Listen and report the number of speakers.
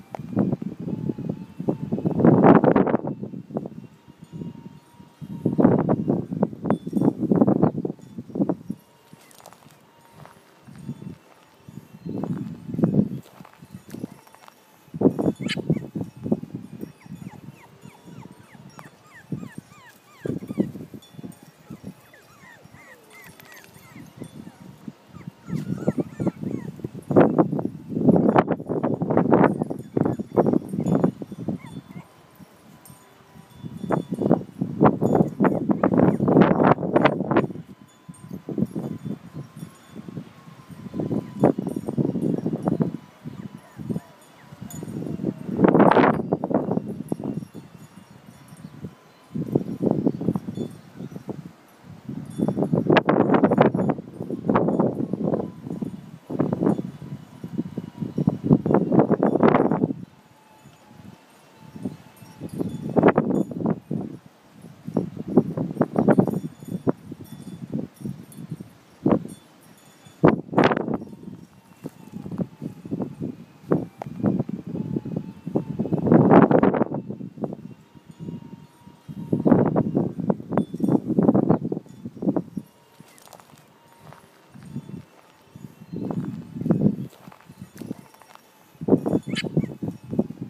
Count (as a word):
zero